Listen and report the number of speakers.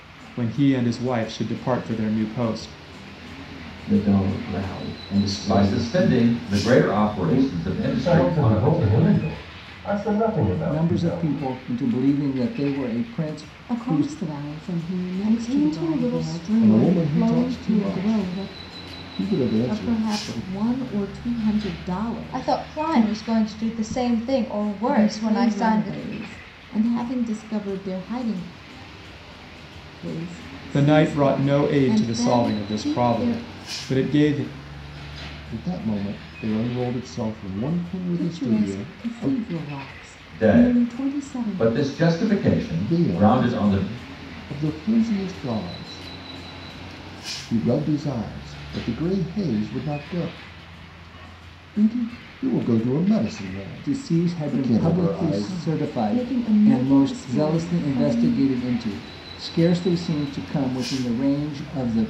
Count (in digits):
10